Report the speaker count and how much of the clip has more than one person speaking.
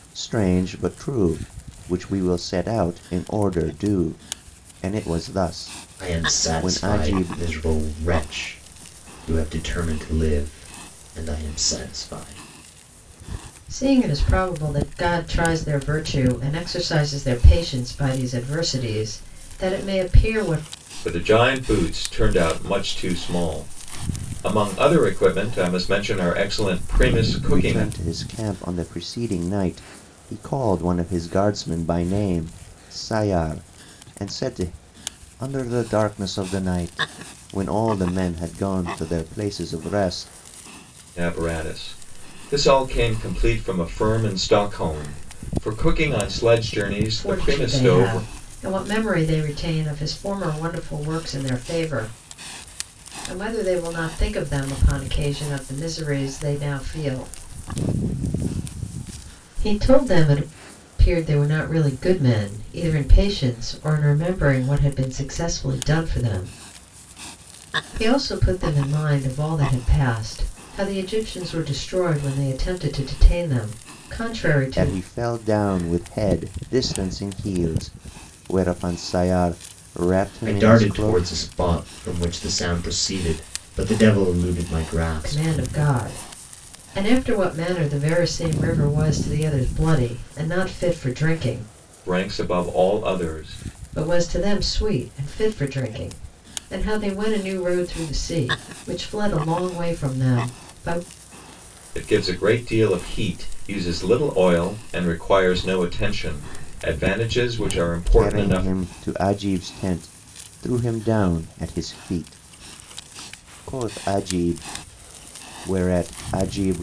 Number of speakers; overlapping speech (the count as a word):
four, about 5%